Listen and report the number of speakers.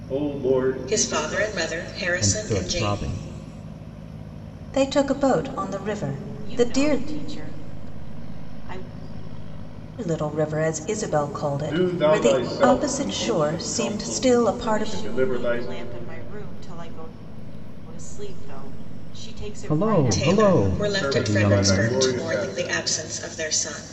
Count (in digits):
5